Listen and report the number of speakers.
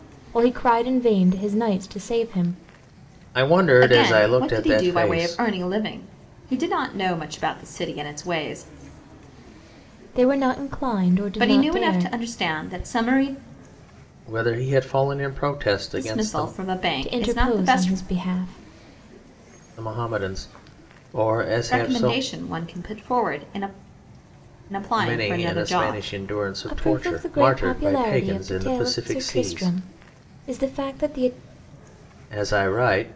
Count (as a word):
three